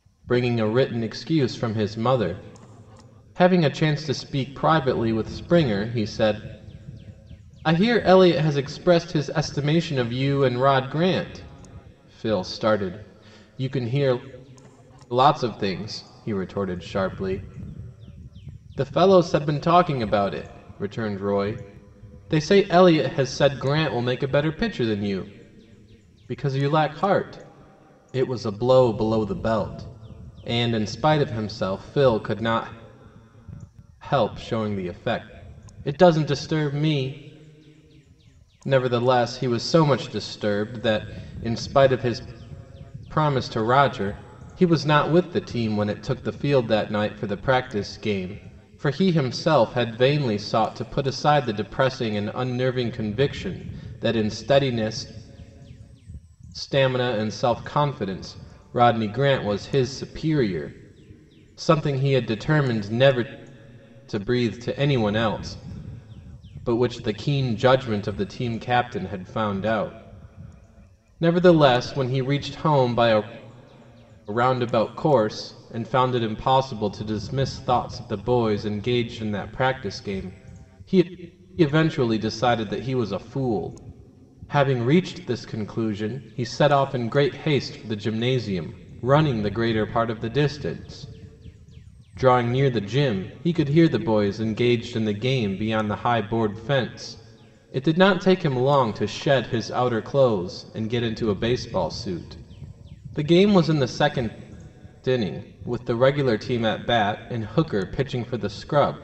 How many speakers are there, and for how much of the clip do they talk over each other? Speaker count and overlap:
1, no overlap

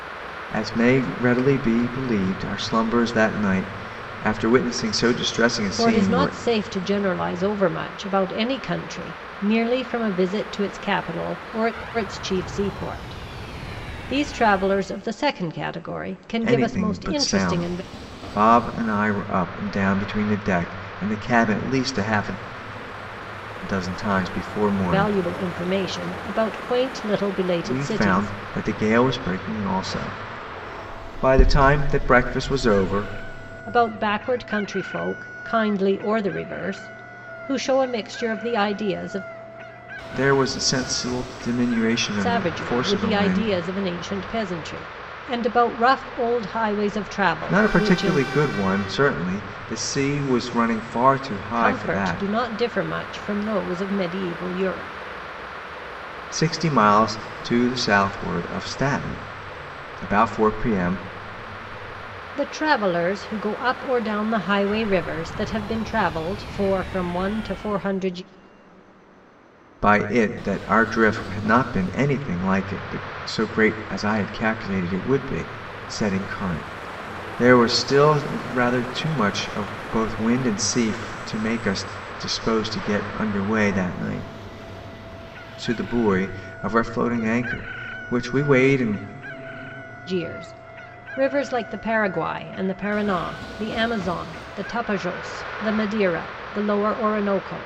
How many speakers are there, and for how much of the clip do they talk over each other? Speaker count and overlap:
2, about 6%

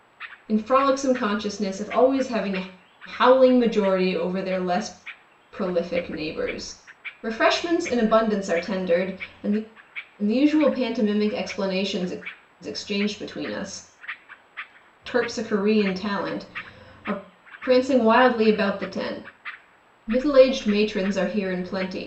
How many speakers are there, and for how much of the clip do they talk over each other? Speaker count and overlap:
1, no overlap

